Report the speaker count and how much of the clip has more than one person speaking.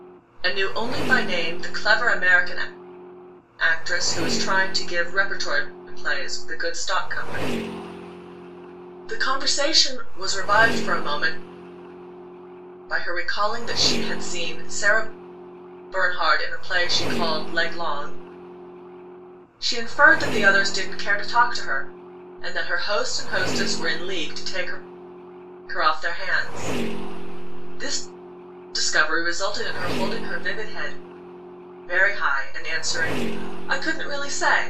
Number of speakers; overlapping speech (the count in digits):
1, no overlap